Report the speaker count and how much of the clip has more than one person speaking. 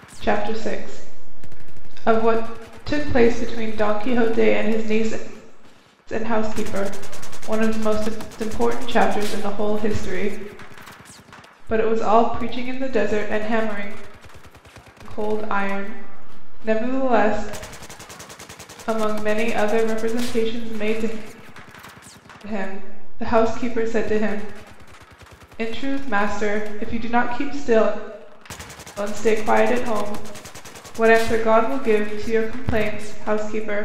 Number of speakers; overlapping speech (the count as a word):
one, no overlap